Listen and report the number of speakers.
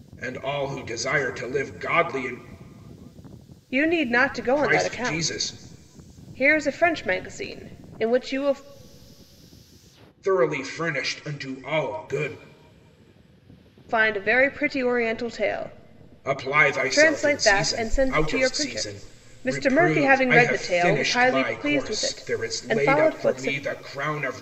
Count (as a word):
two